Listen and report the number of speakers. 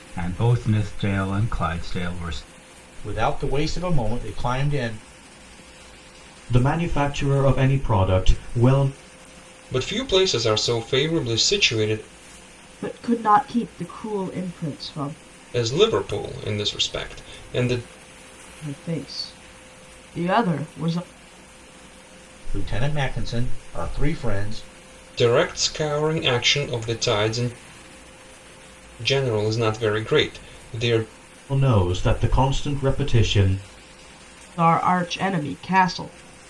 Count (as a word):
five